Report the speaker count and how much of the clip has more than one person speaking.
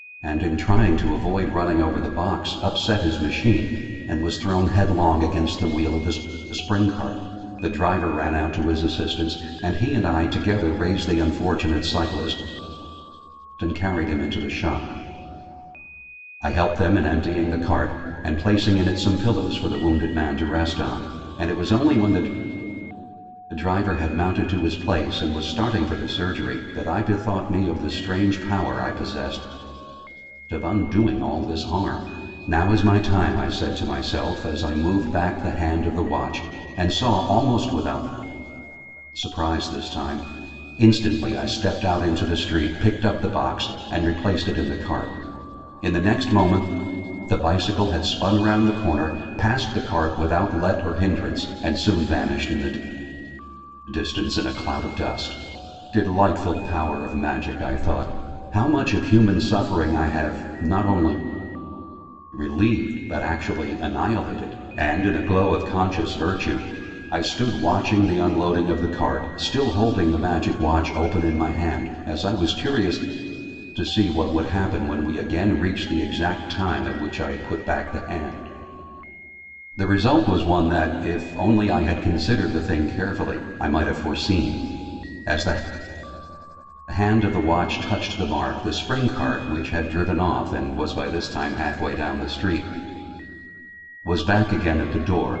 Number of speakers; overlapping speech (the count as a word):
one, no overlap